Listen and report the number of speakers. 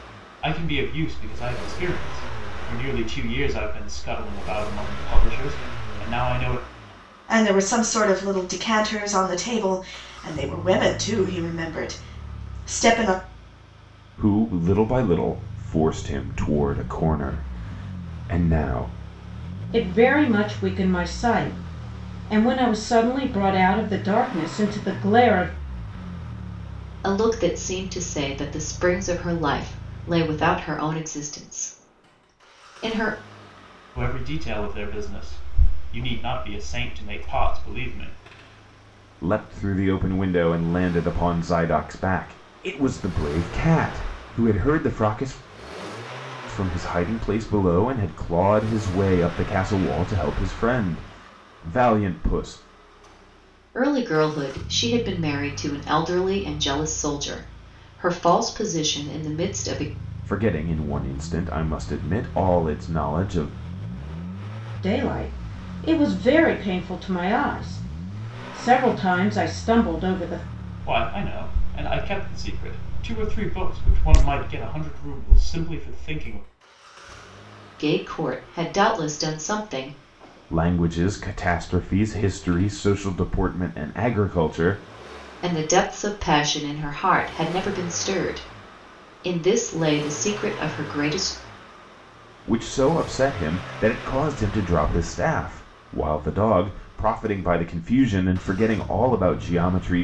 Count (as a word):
five